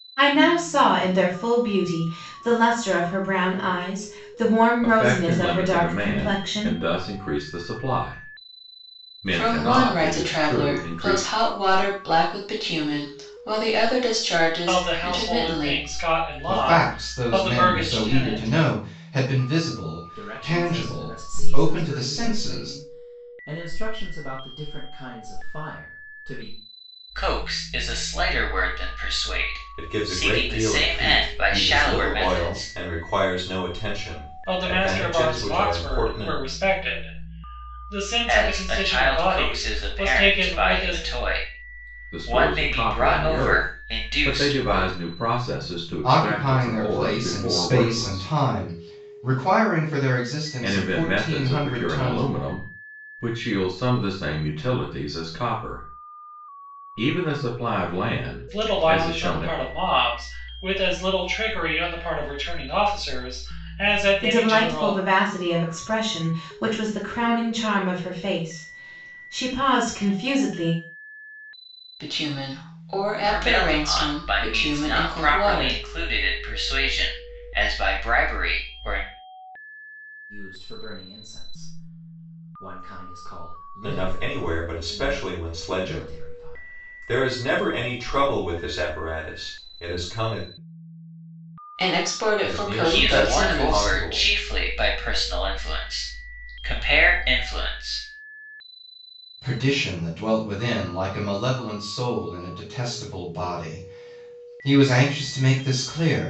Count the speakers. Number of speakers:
8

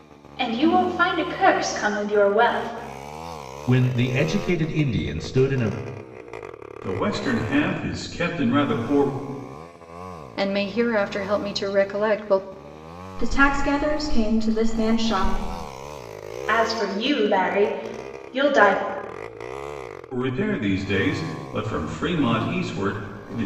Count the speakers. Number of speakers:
5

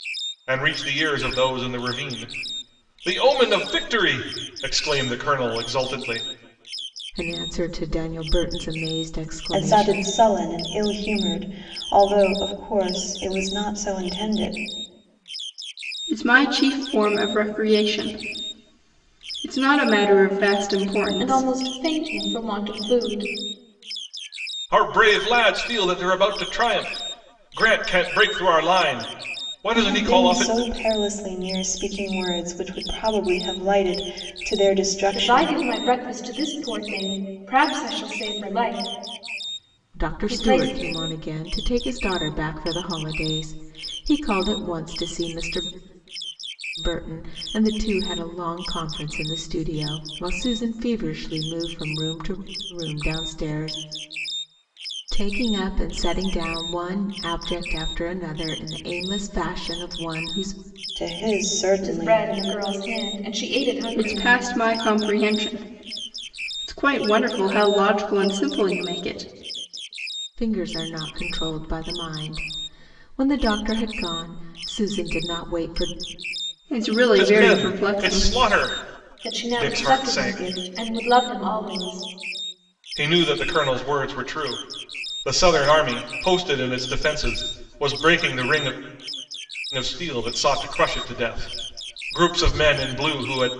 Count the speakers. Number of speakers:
5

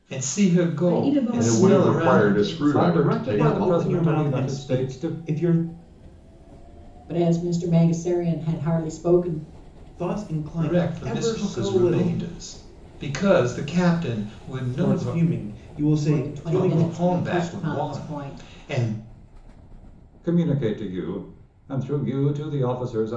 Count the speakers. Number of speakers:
6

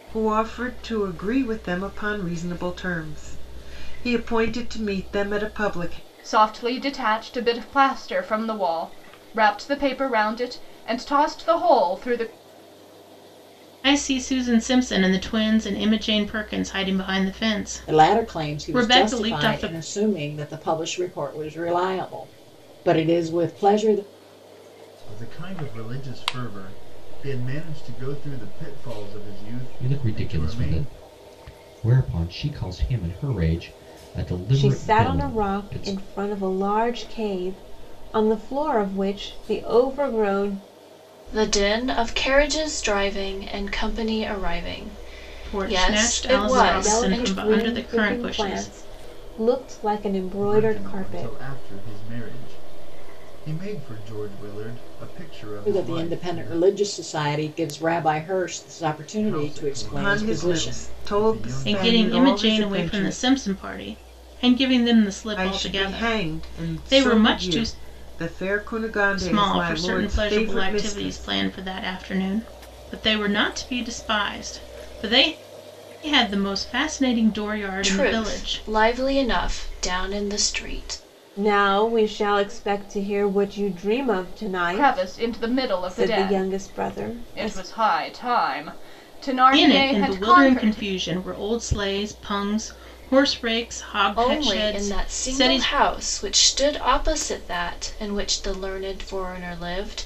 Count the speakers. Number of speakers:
8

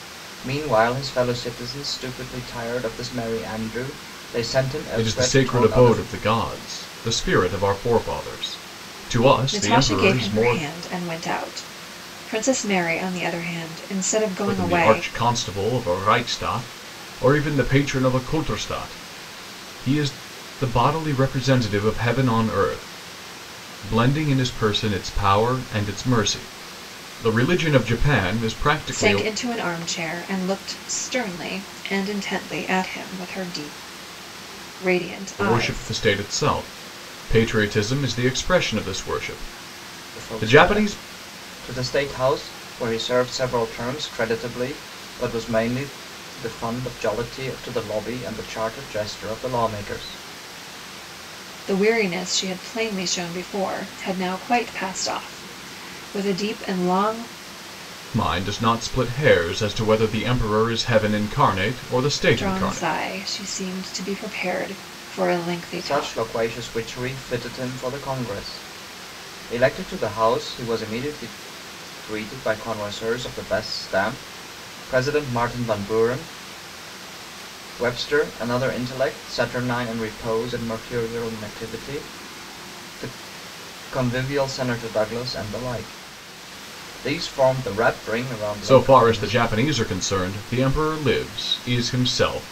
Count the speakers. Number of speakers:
3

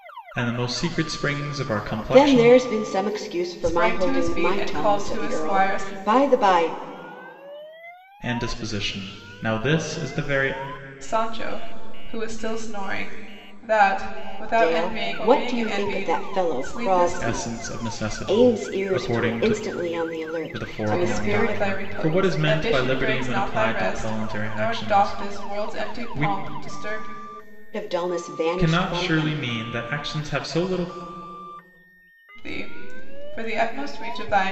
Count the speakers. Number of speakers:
3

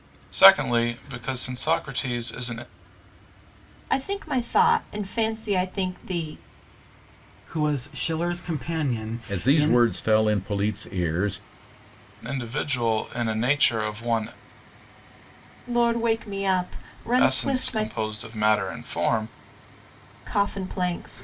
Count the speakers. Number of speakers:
4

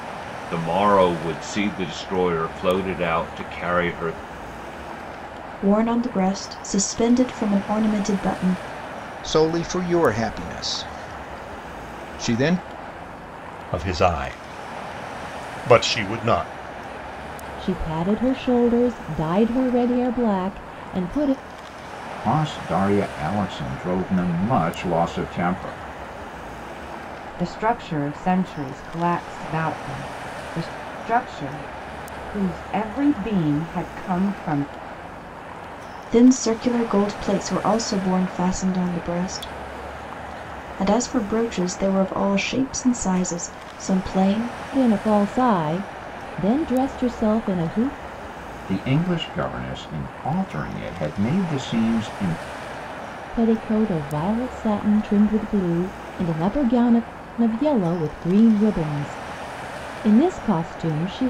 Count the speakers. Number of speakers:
7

